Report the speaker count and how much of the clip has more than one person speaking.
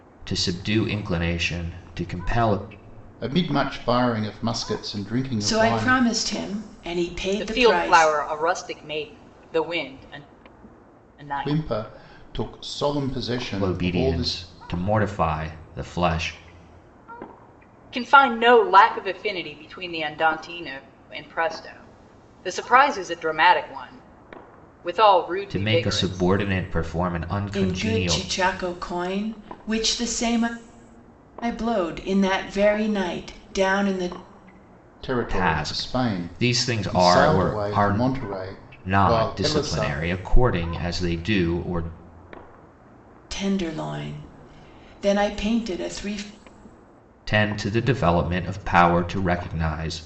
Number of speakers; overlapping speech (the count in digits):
4, about 15%